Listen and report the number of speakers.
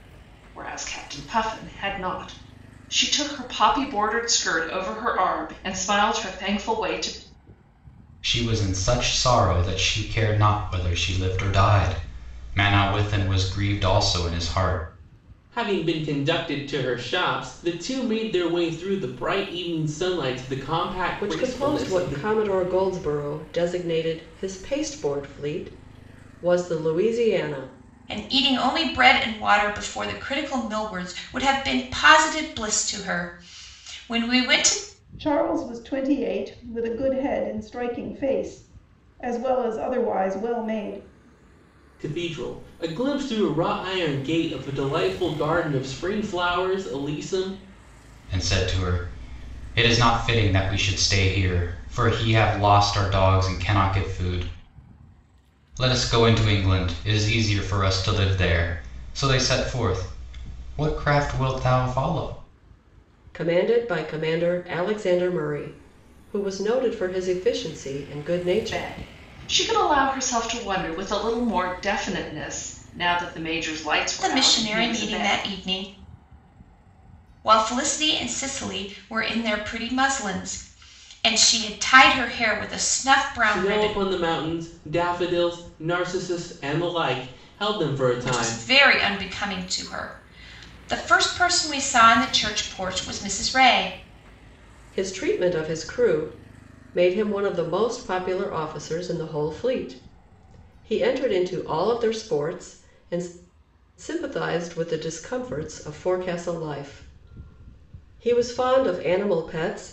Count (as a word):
six